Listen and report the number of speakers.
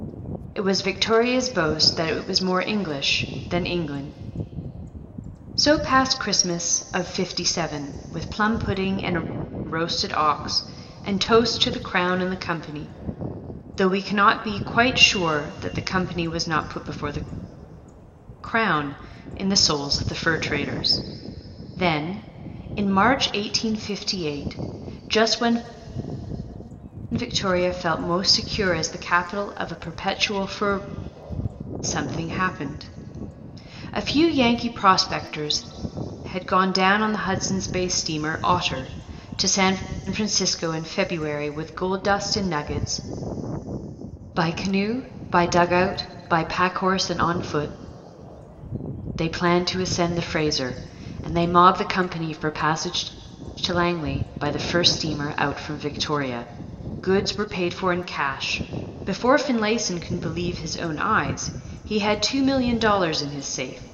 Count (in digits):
1